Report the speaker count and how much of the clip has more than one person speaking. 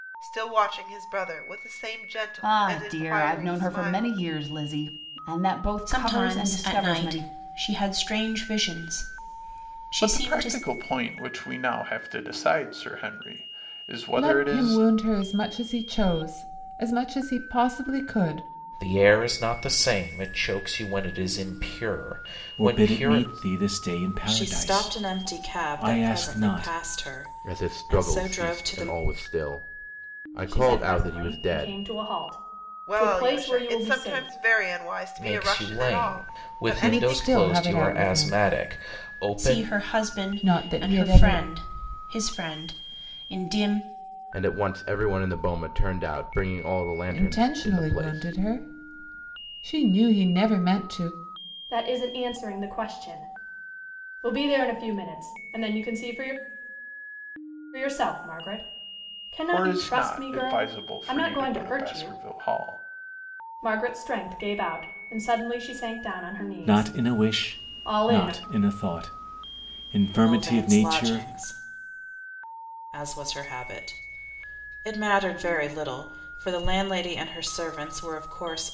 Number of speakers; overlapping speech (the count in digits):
10, about 32%